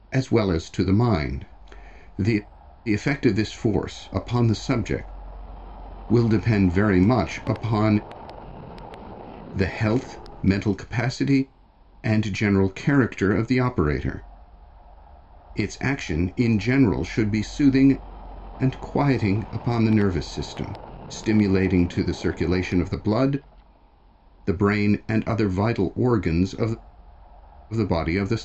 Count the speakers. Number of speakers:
1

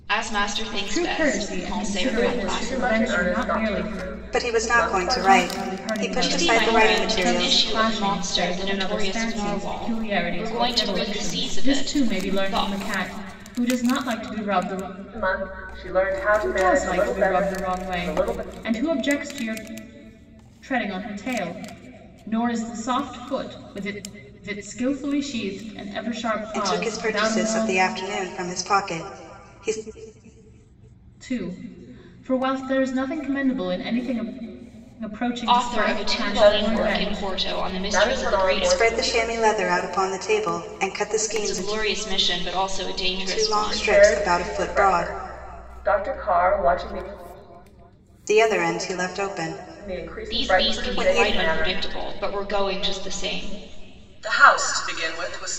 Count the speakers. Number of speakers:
4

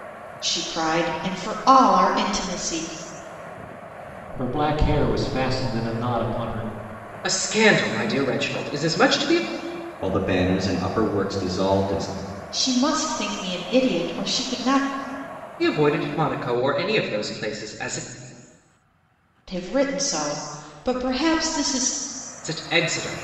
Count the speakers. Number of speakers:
4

